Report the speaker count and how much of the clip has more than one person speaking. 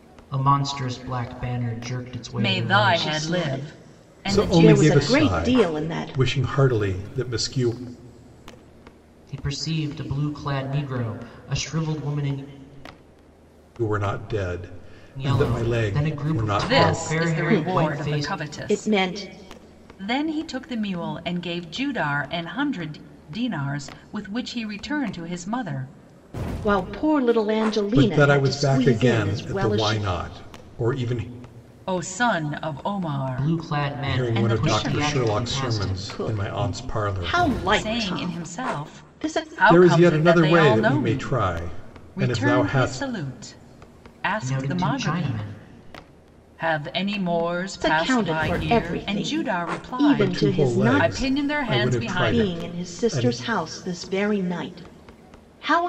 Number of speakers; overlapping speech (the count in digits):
4, about 44%